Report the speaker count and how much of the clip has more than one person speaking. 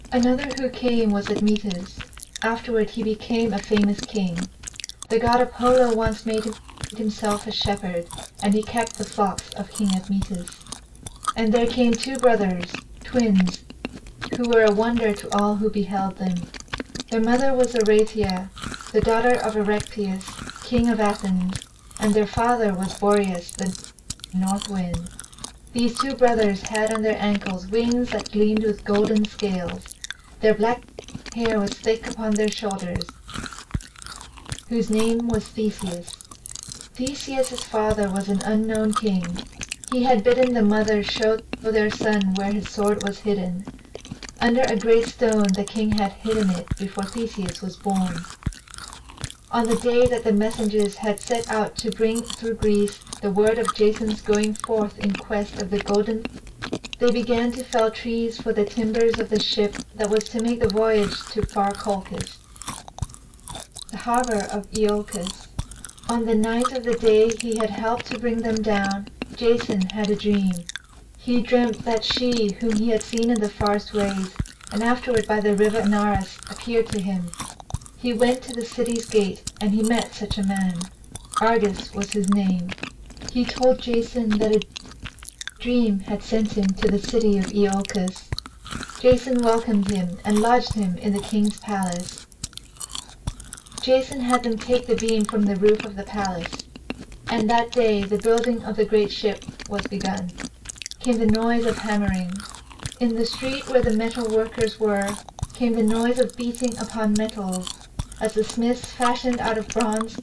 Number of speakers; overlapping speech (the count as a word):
one, no overlap